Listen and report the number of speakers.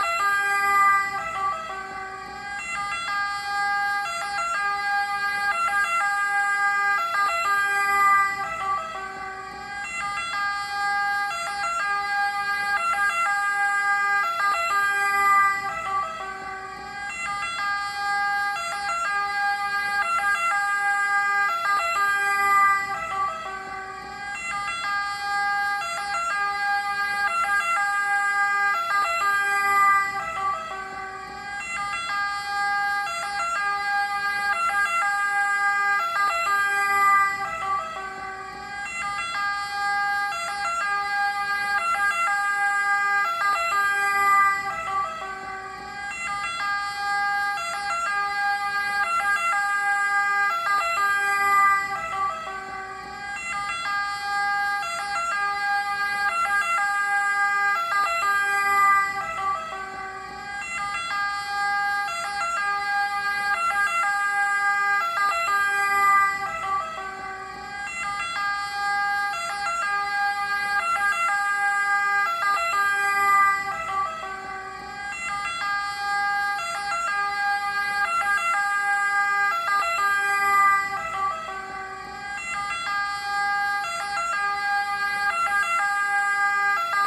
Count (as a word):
zero